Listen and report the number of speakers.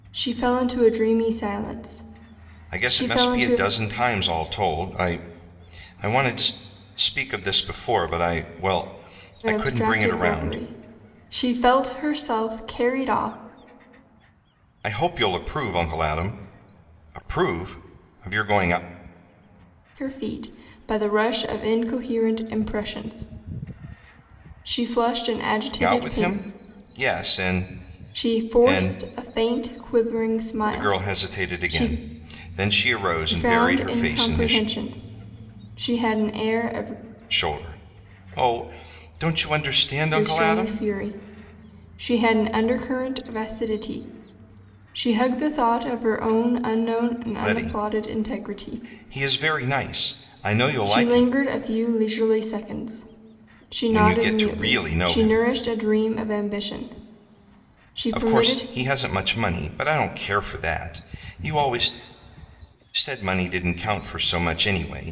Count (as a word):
two